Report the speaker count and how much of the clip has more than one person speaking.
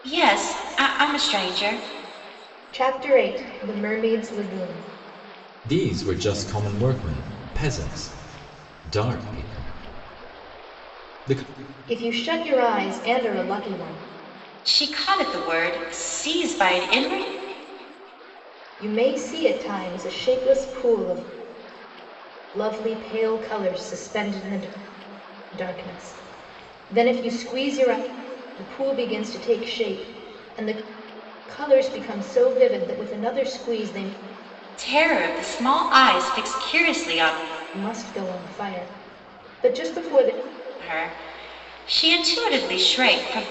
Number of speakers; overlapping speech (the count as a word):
three, no overlap